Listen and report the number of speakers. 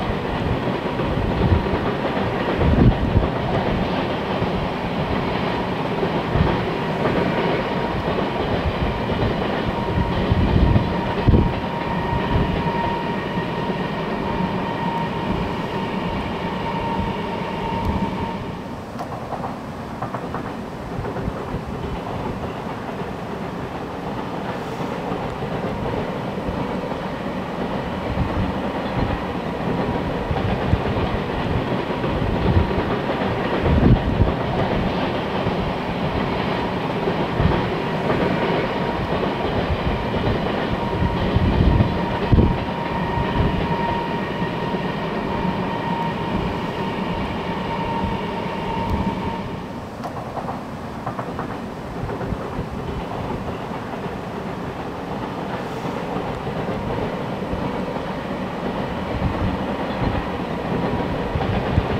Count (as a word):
zero